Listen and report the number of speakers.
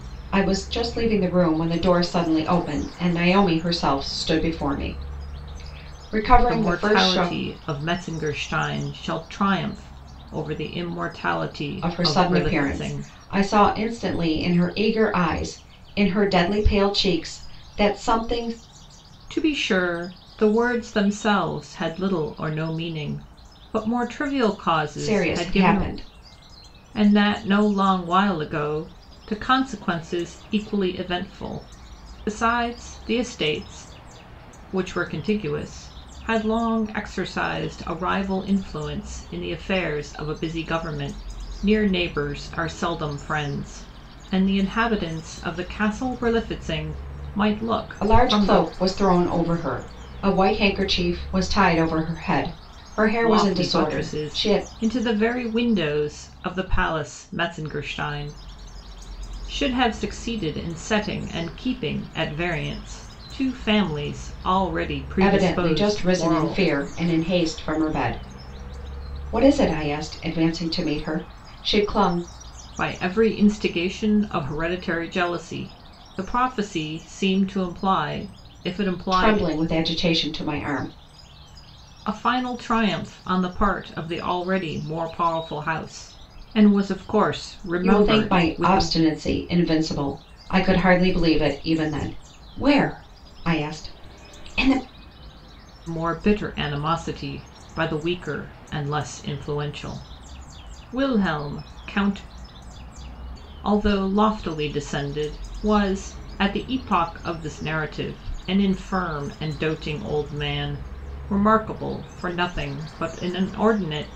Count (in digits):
2